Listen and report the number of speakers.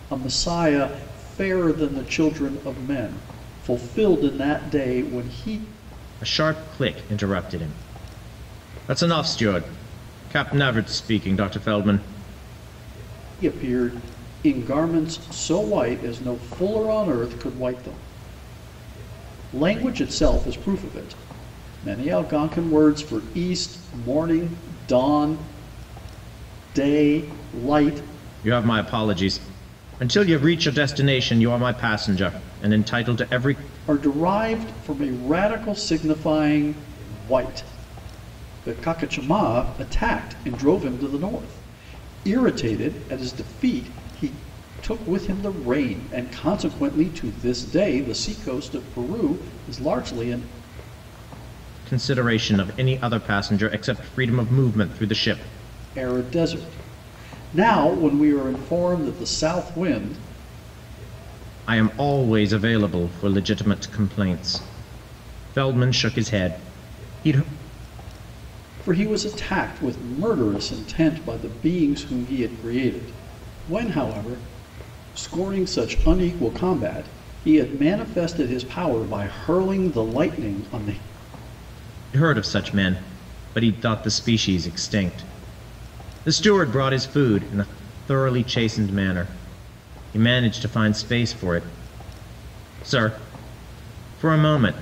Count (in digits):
2